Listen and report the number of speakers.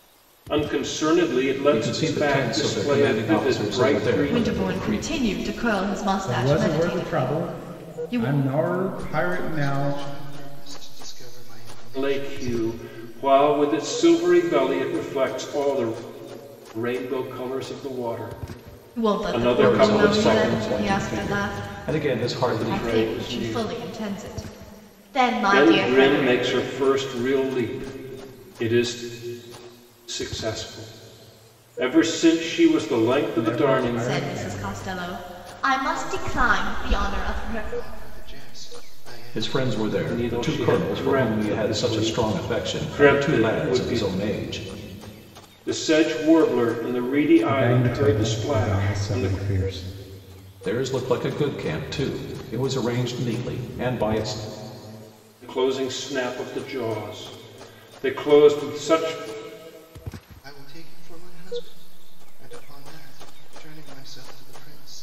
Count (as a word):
five